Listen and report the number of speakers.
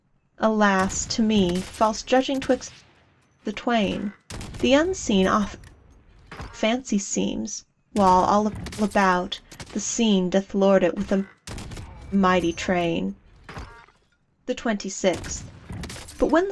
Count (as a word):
one